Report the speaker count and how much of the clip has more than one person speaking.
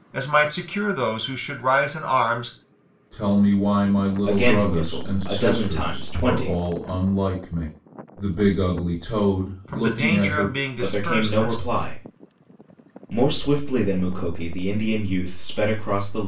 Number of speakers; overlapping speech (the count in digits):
3, about 26%